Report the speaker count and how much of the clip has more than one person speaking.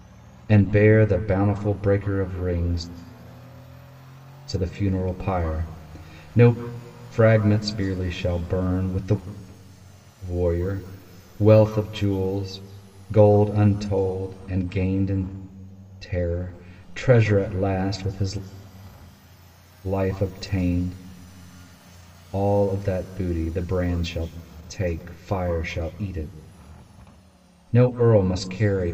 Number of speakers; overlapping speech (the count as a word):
one, no overlap